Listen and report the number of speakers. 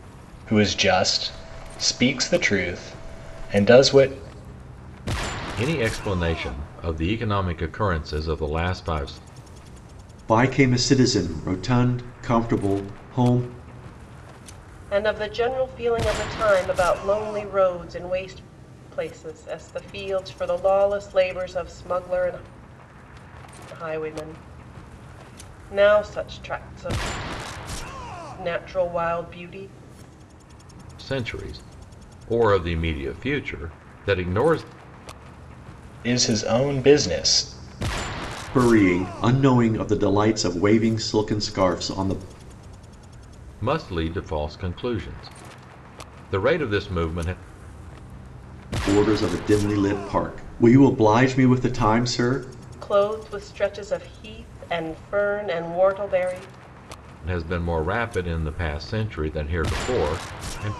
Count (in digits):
4